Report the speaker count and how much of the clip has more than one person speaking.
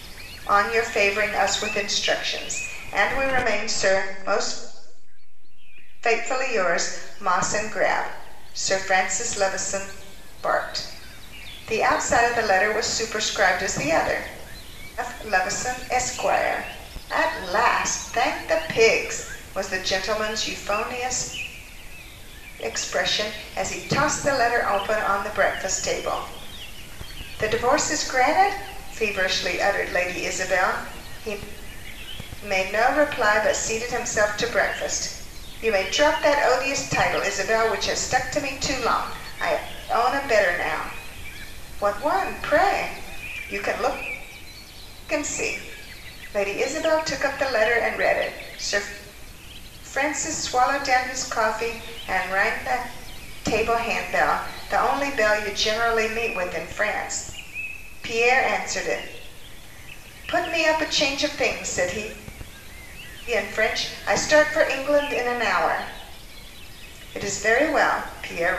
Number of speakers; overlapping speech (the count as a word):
one, no overlap